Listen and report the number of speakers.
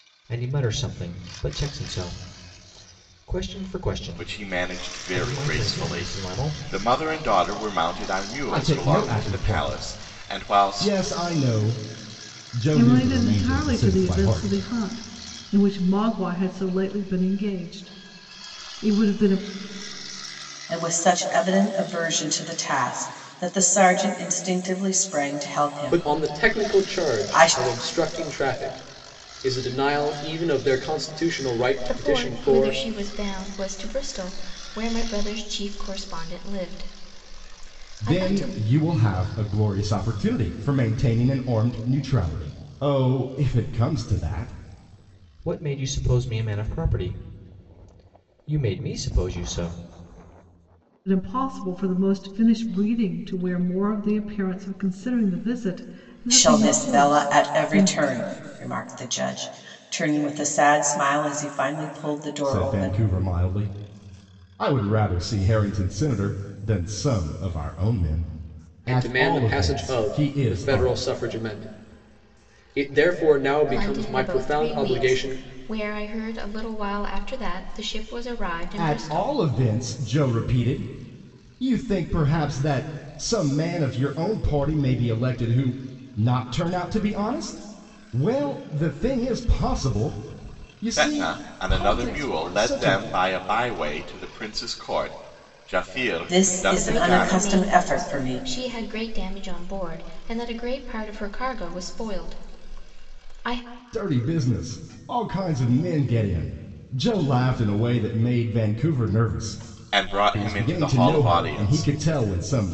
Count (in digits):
7